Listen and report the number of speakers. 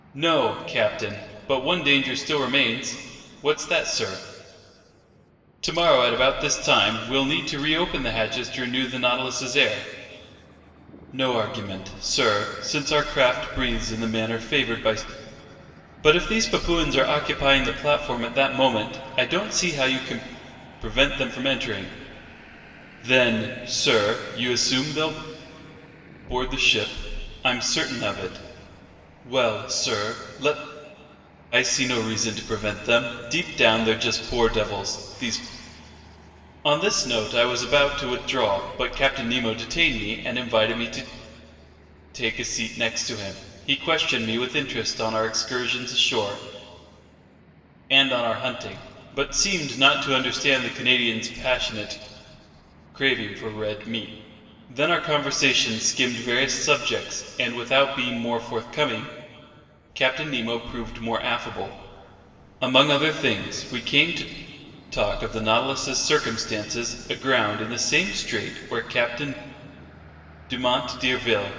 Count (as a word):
one